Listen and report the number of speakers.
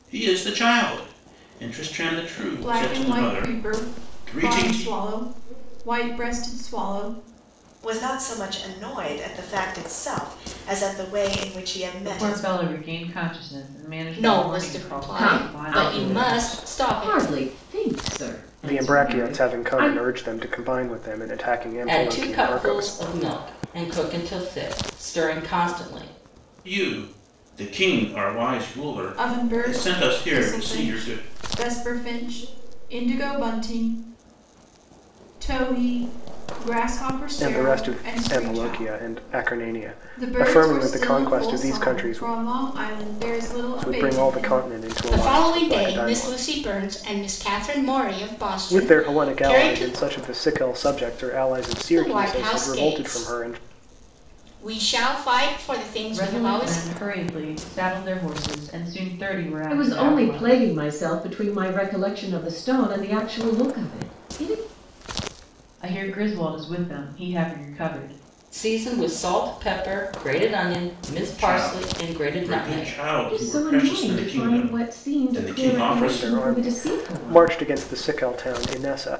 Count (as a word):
eight